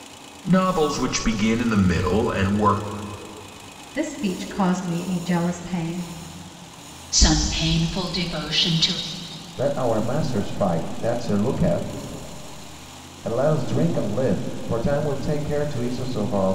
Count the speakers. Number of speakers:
four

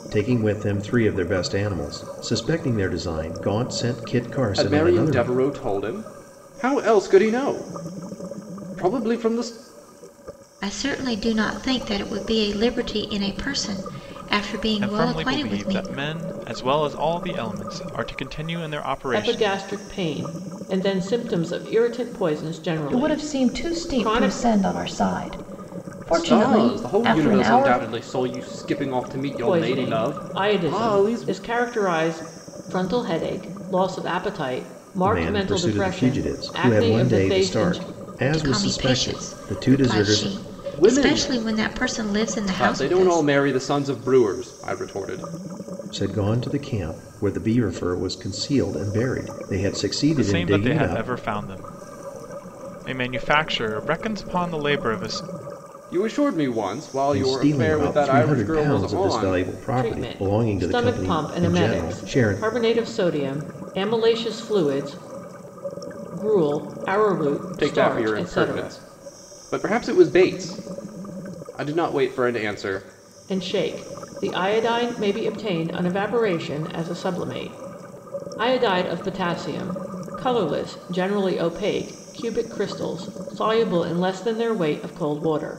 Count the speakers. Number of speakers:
six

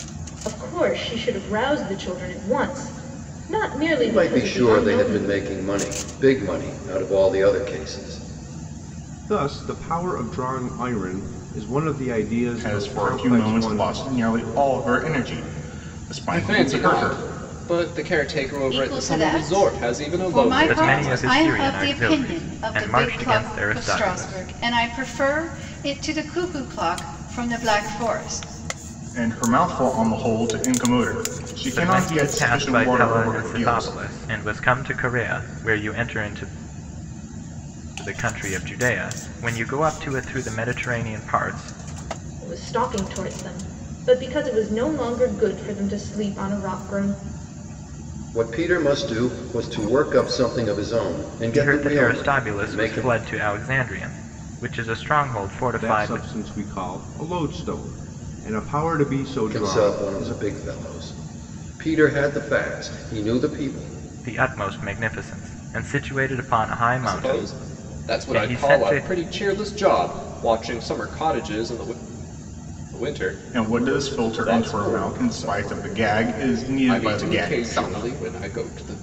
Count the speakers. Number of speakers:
seven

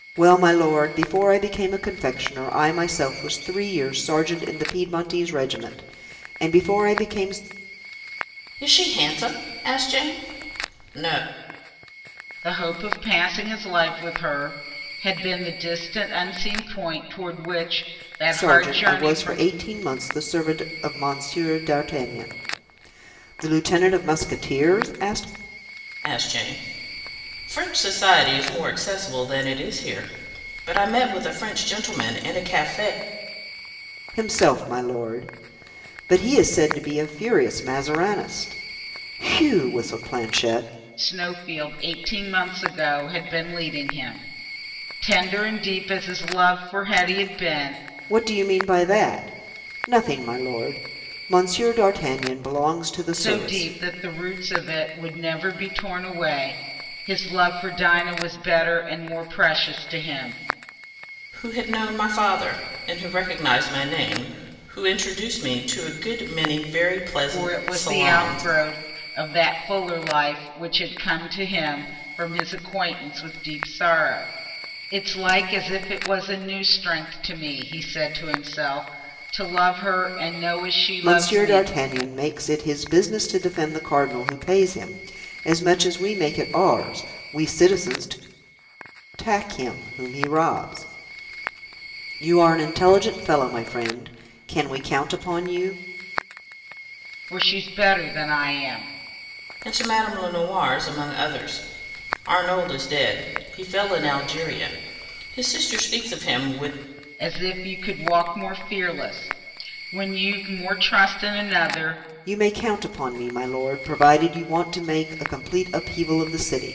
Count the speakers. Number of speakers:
three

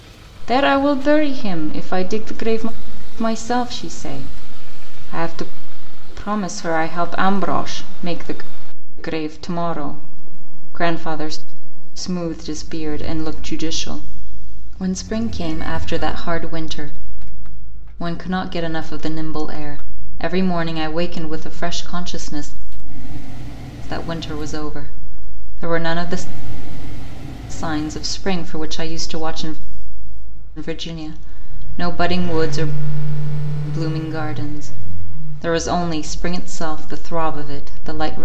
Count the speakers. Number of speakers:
one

